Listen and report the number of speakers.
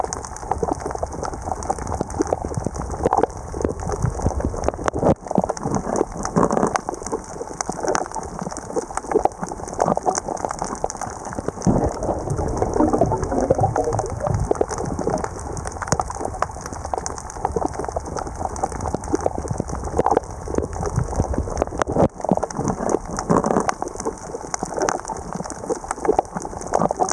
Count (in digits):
0